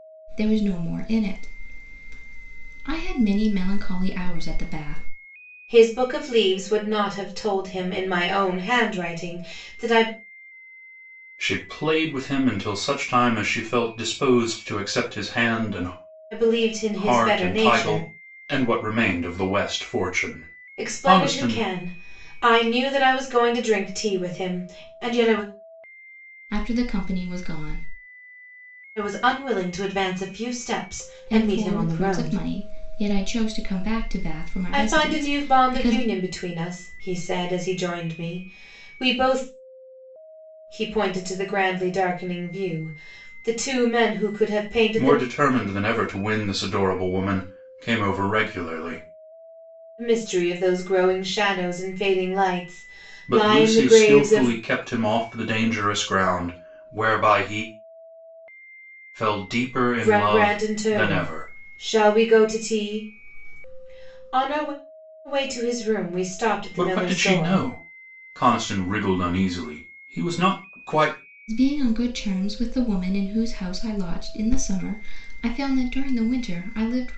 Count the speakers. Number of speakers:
3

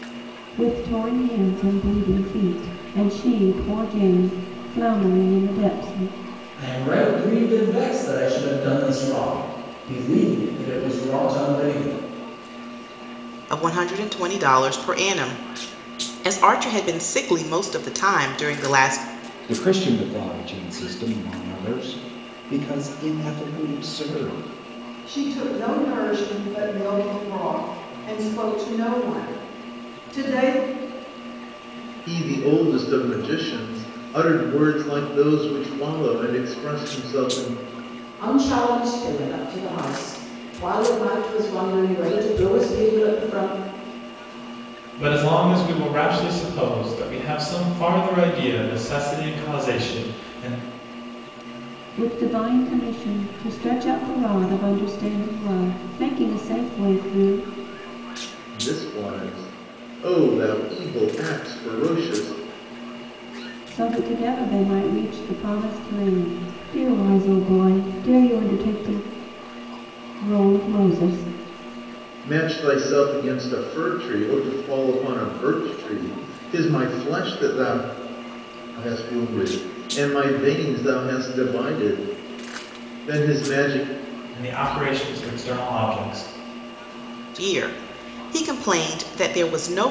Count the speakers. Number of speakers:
8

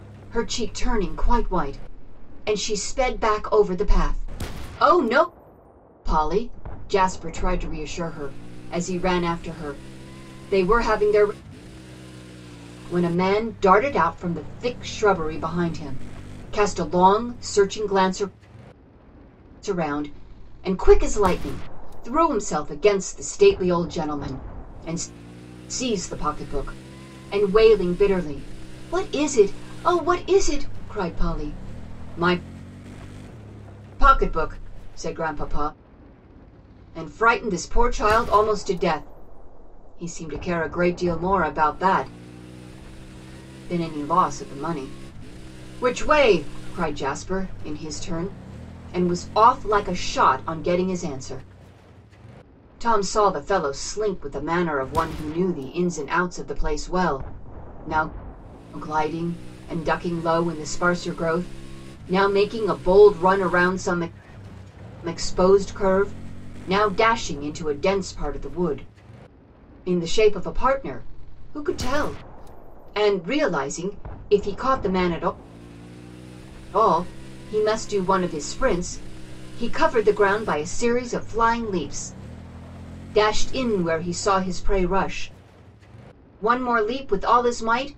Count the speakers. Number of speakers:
1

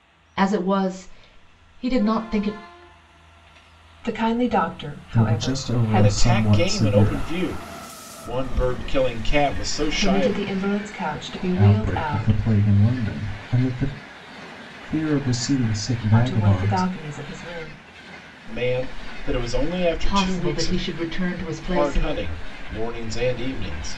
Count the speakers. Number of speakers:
4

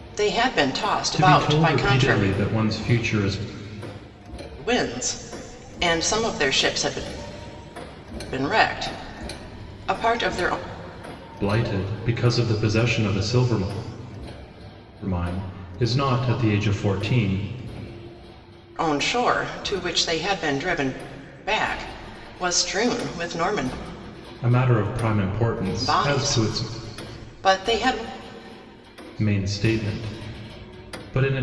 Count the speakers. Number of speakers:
2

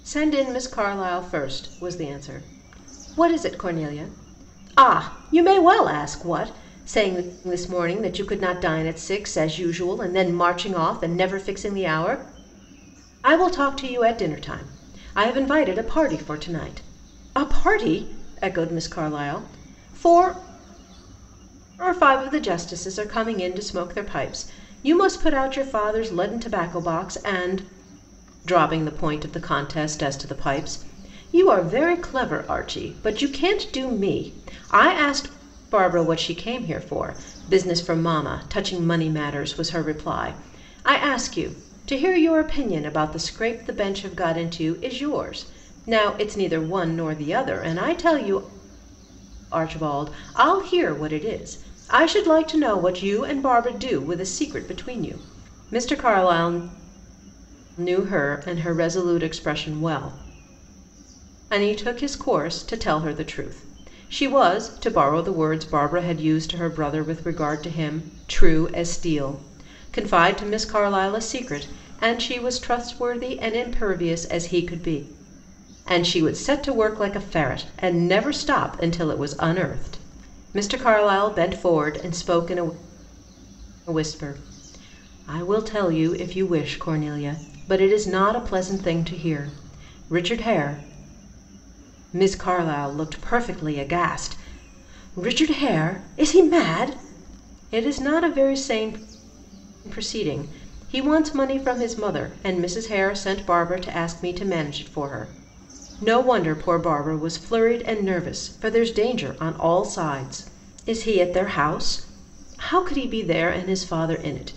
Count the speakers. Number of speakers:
1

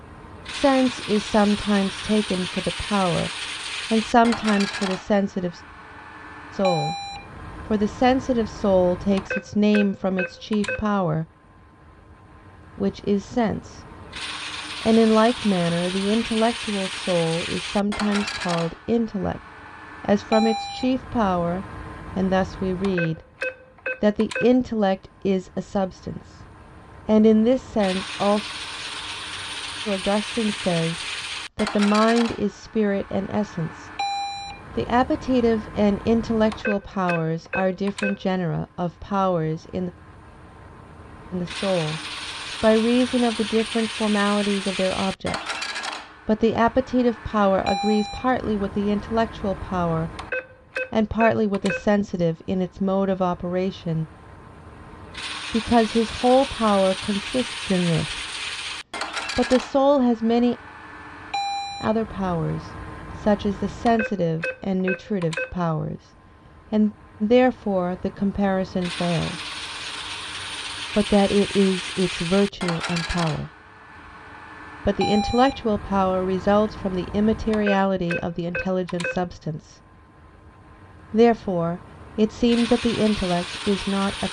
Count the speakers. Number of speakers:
1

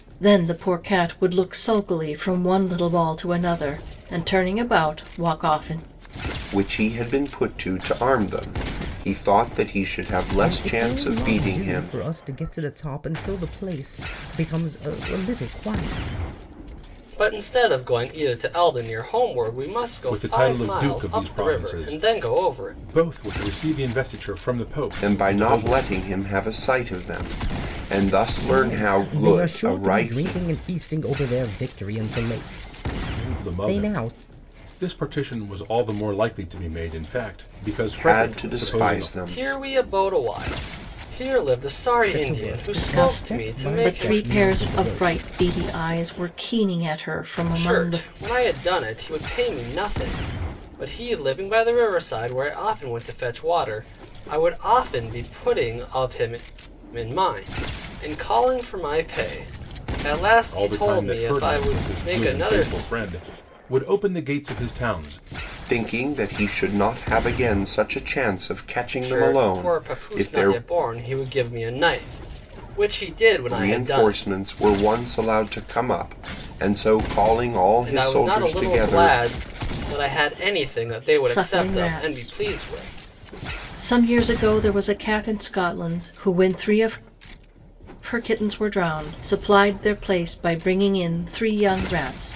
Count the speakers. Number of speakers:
5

